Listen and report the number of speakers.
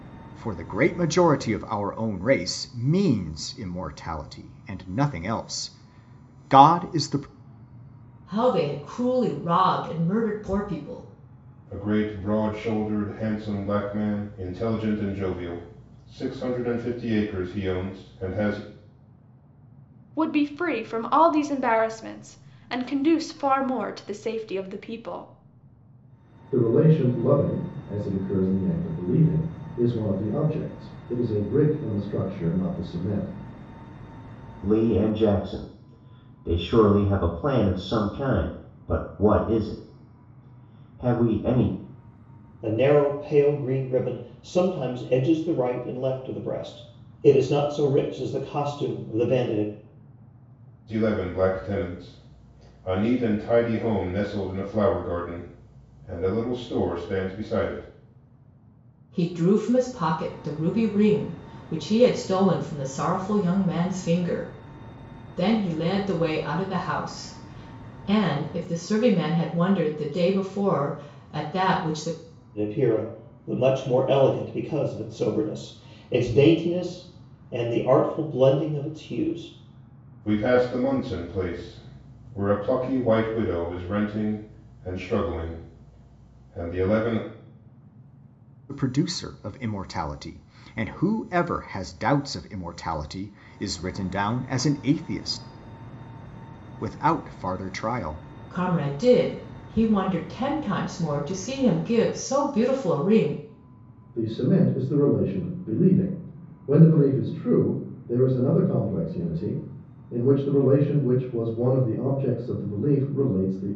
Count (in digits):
7